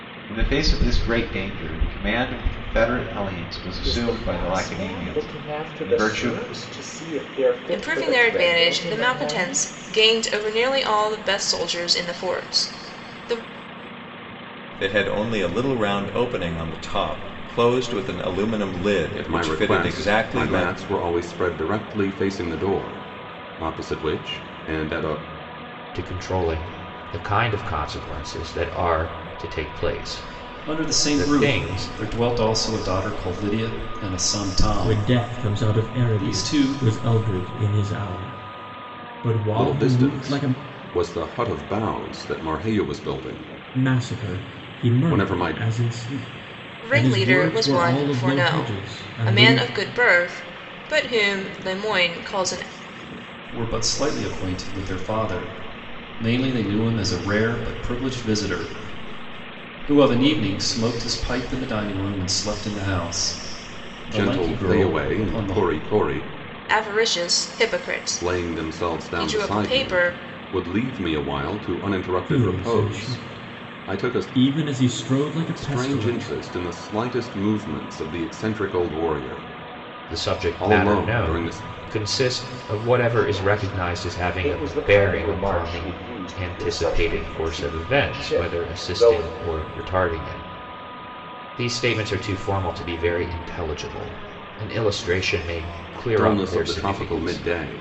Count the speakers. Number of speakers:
8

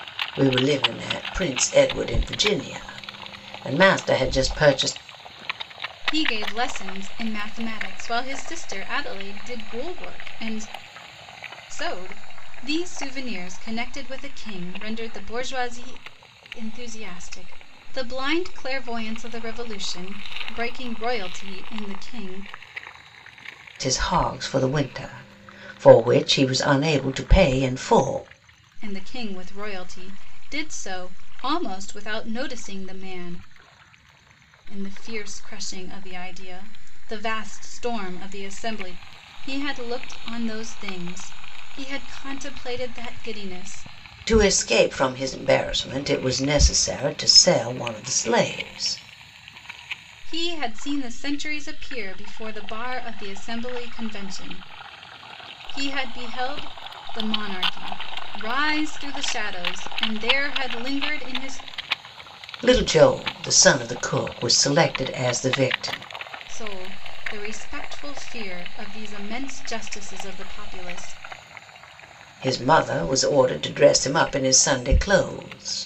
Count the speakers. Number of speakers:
2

